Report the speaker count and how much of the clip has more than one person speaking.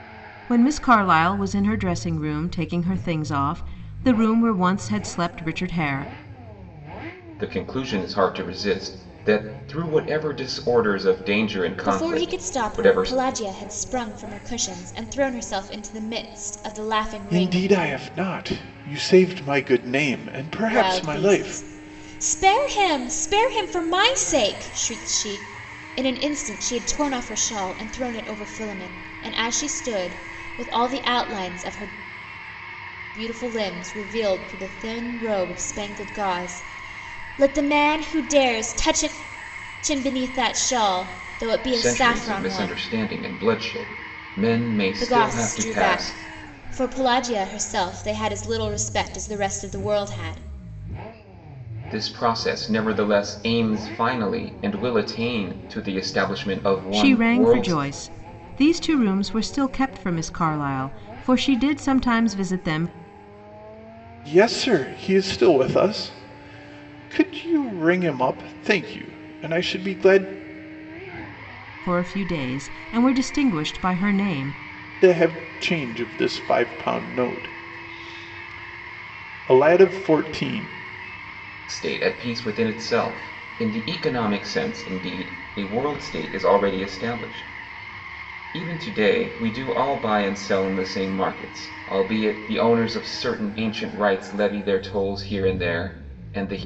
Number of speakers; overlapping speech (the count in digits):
4, about 6%